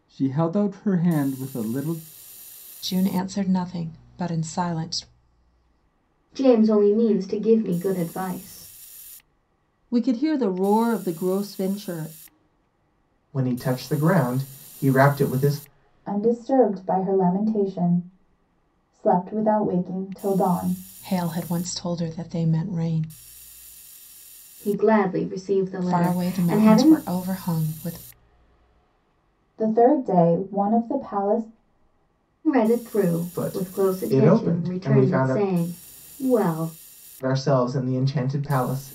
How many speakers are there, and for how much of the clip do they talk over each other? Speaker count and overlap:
6, about 9%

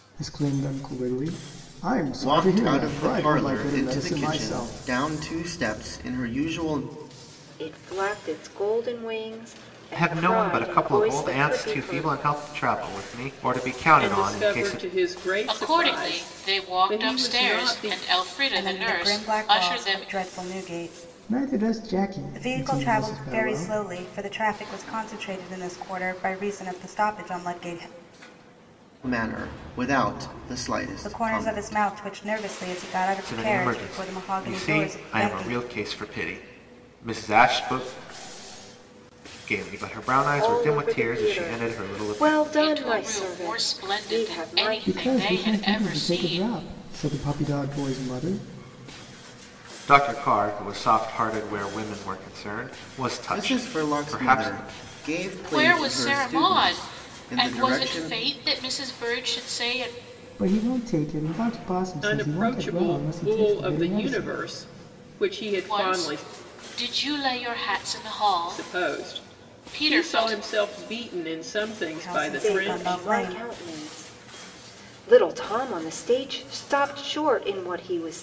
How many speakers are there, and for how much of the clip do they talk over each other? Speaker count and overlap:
7, about 41%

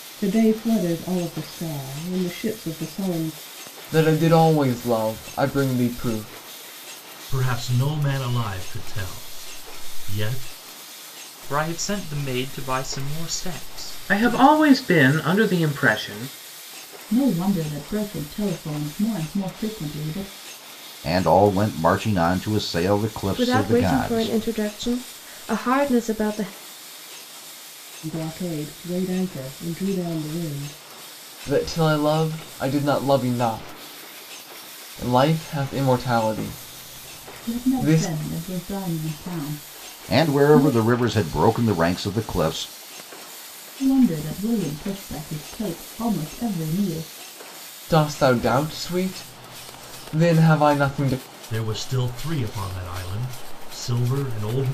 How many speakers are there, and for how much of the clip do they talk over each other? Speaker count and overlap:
8, about 5%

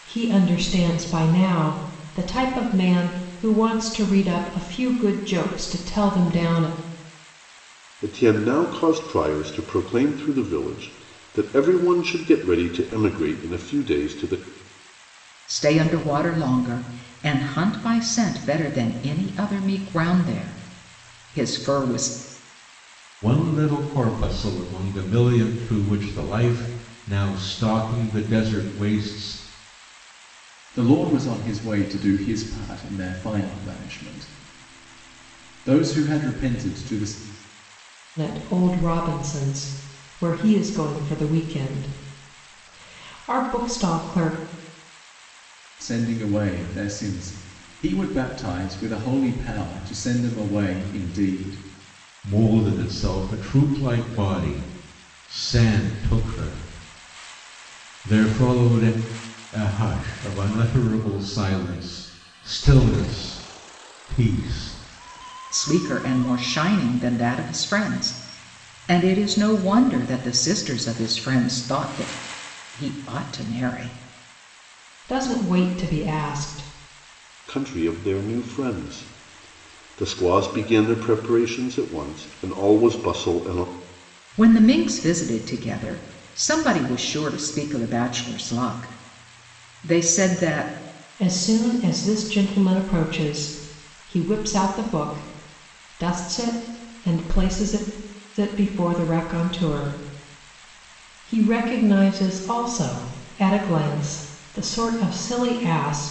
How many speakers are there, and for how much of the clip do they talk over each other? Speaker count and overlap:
5, no overlap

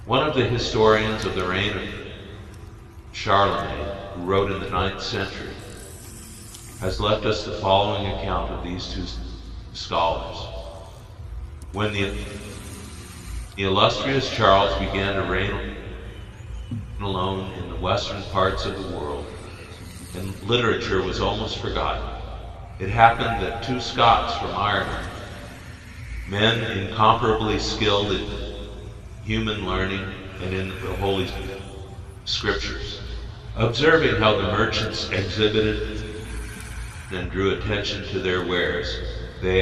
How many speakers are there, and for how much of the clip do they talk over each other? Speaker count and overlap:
1, no overlap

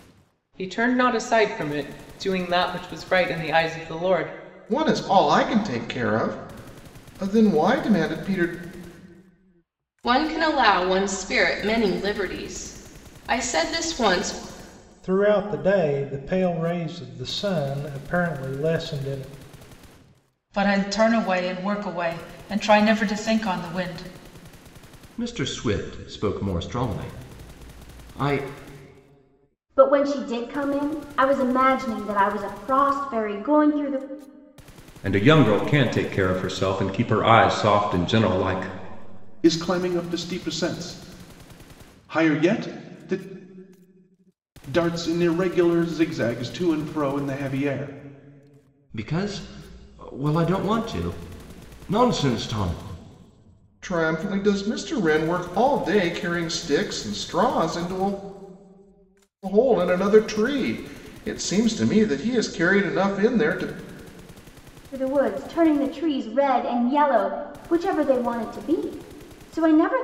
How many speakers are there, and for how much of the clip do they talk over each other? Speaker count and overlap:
9, no overlap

